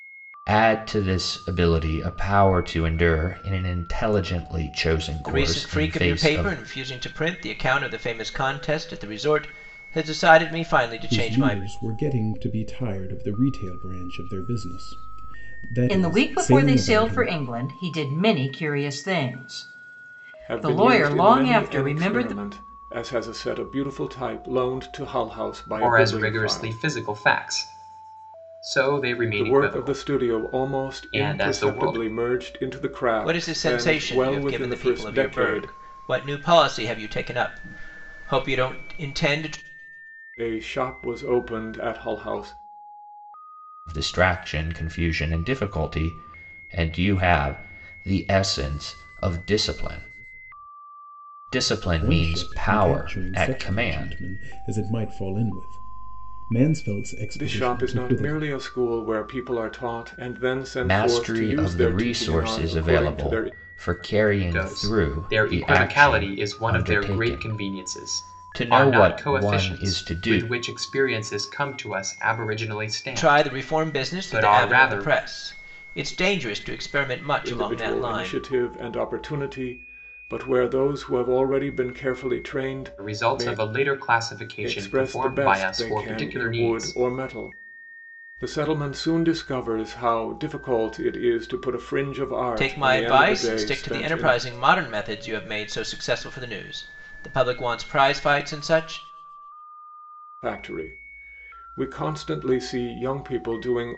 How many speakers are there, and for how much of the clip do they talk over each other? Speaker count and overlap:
six, about 30%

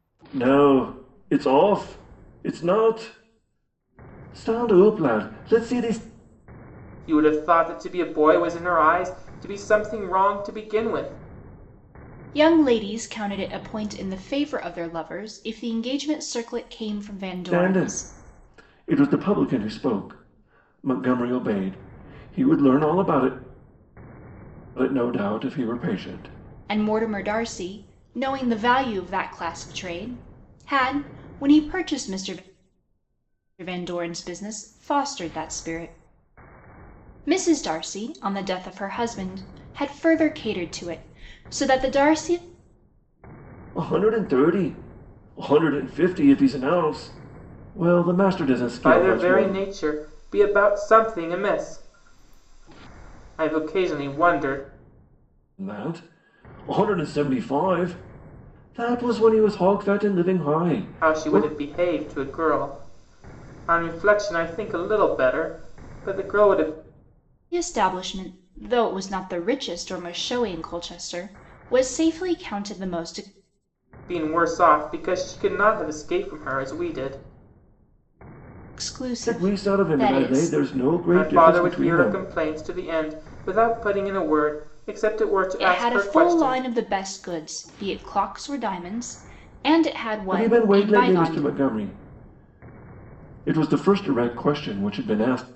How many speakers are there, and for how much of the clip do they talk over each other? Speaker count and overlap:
three, about 7%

